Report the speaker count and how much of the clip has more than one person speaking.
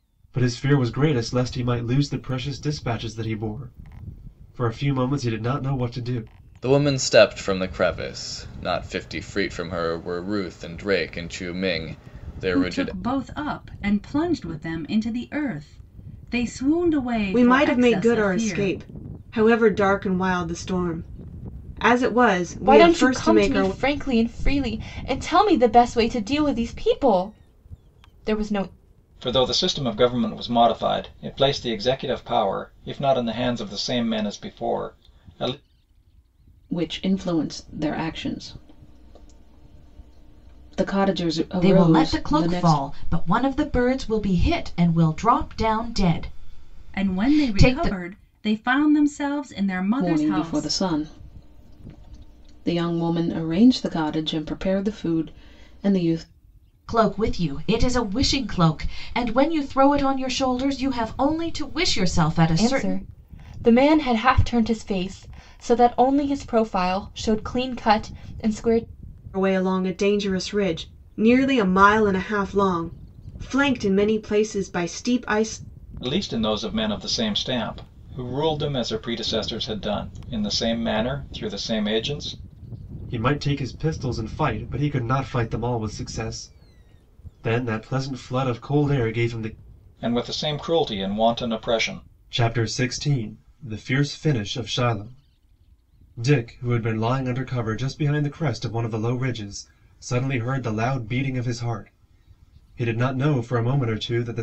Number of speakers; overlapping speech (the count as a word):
eight, about 7%